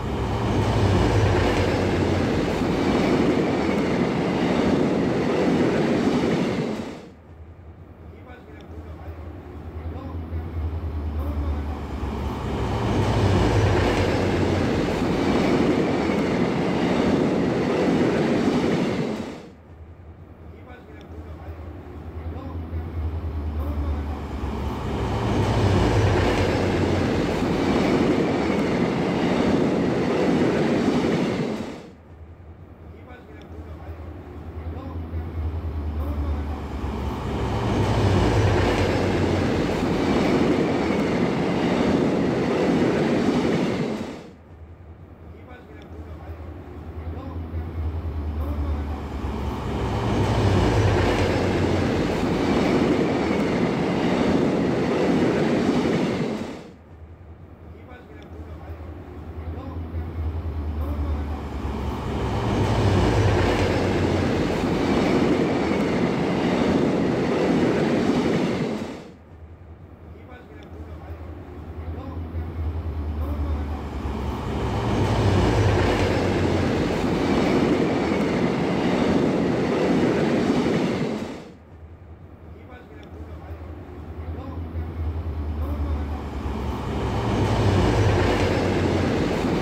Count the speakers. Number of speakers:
zero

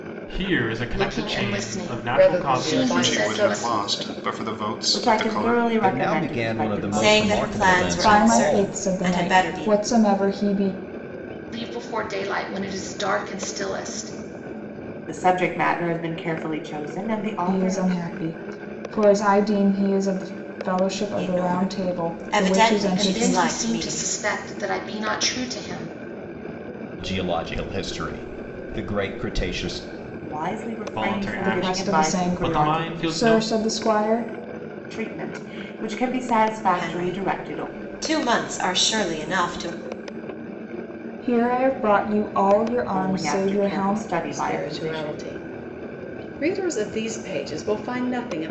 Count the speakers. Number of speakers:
eight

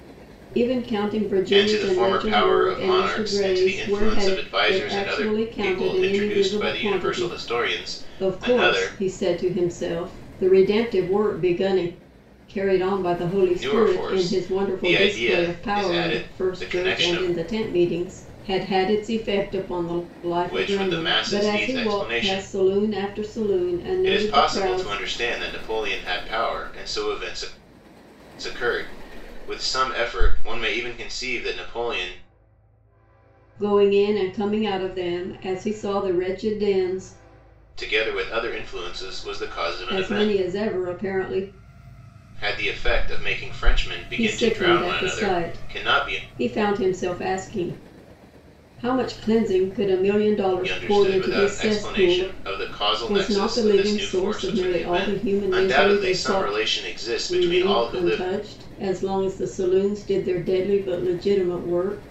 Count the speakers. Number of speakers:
two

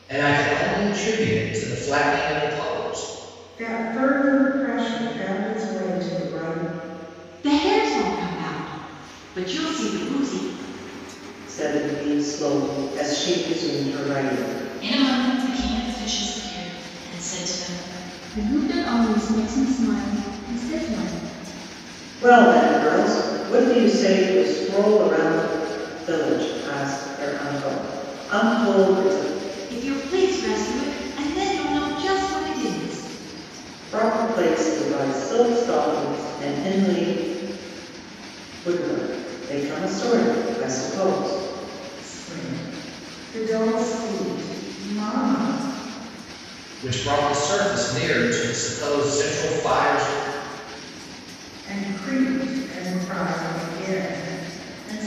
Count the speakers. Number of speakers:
six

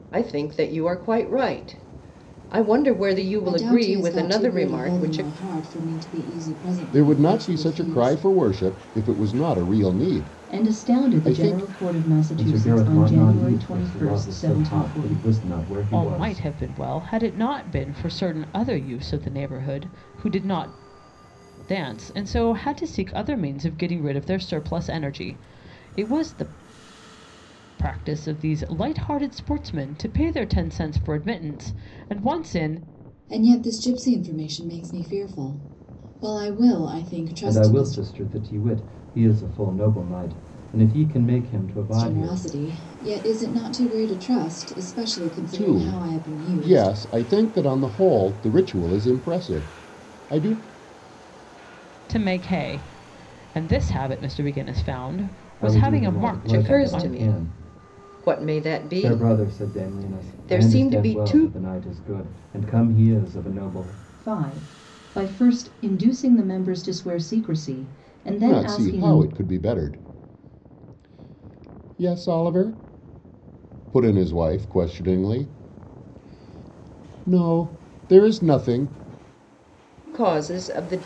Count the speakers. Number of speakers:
six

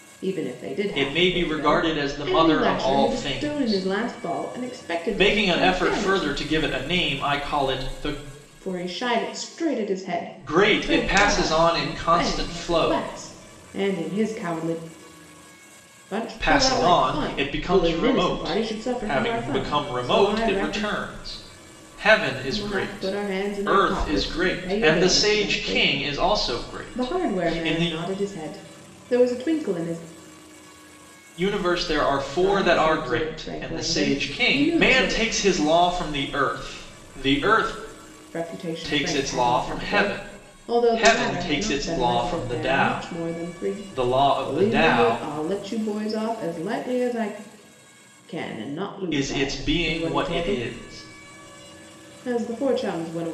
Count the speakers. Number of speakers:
two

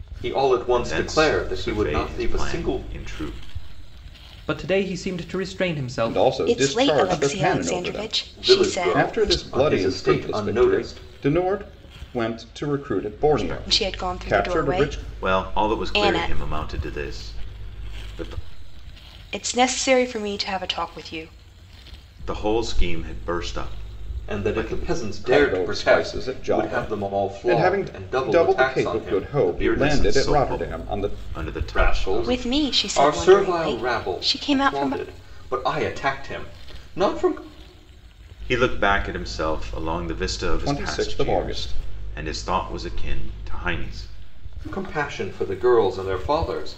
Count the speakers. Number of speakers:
five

